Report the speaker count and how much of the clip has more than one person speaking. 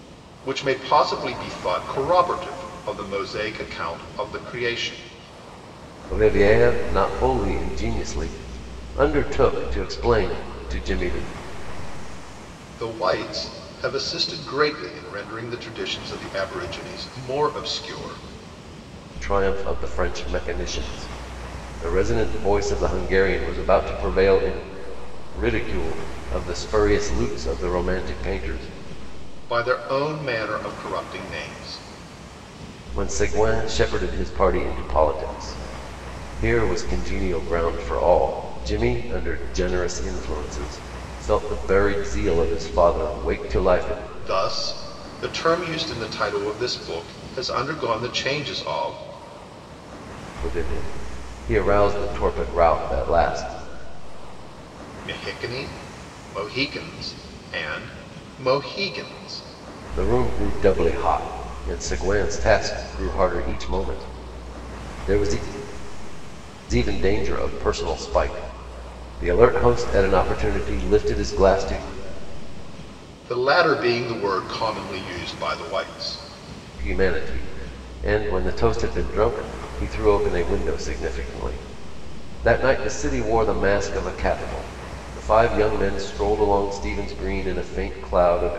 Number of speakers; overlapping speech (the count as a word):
two, no overlap